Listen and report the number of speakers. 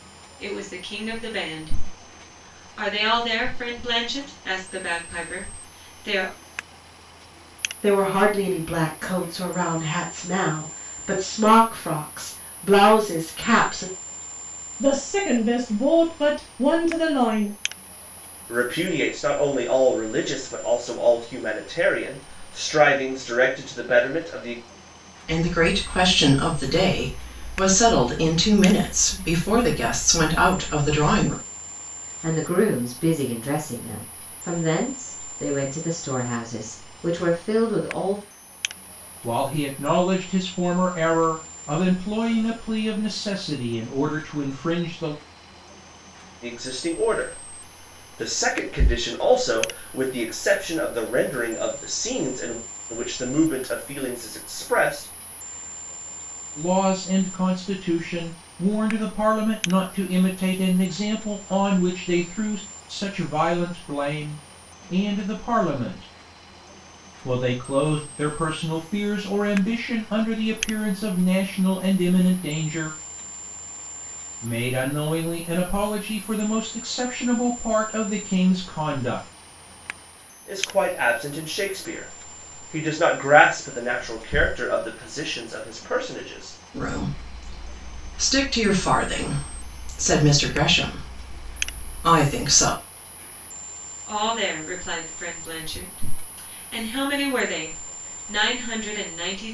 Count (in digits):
7